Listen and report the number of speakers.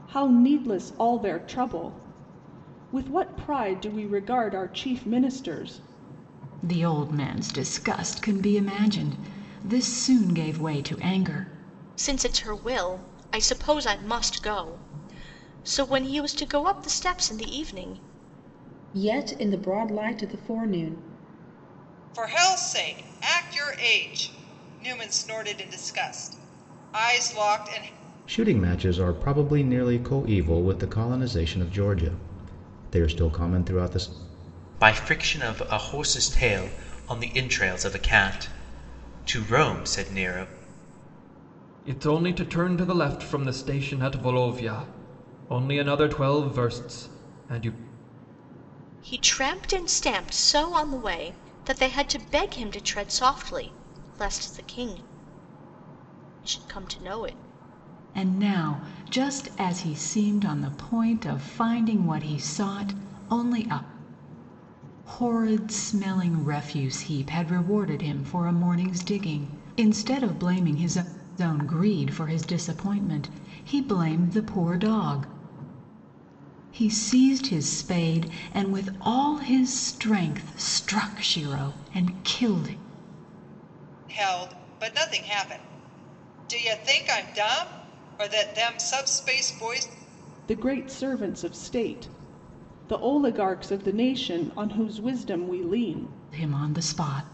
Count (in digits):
8